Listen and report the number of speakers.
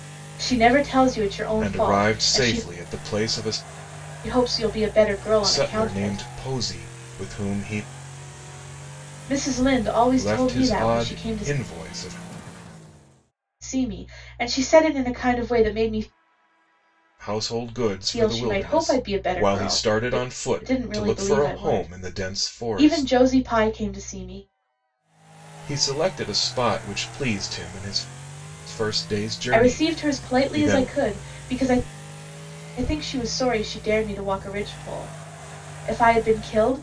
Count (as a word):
two